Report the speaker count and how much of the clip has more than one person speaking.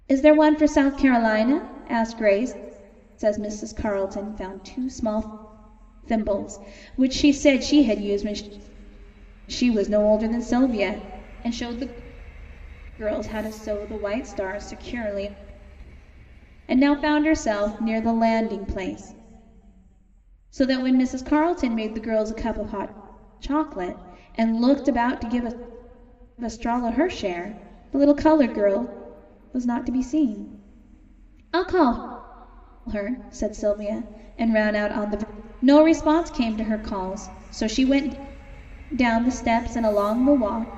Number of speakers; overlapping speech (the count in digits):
1, no overlap